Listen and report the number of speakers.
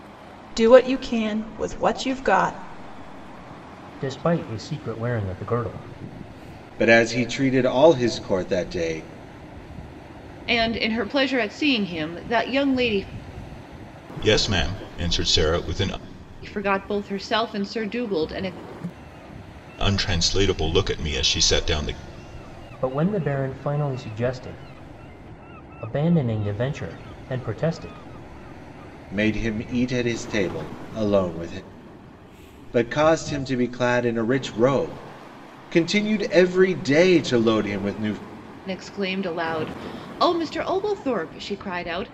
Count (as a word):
five